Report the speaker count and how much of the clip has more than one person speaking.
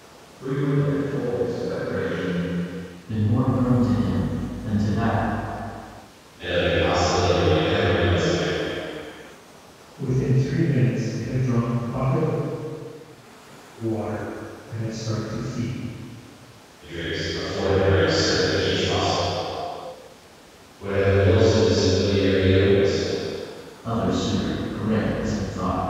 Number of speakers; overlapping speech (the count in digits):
4, no overlap